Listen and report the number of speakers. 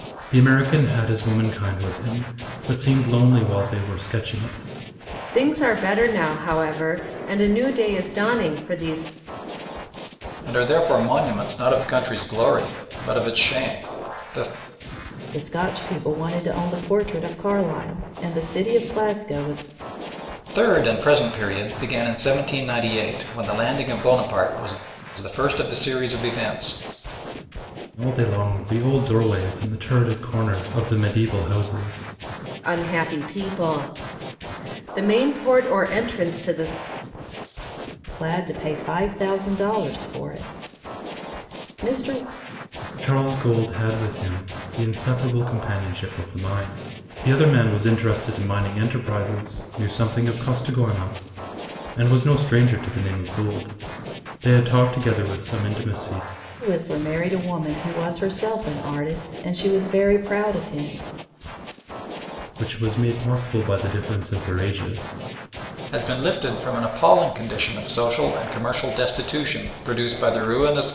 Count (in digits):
4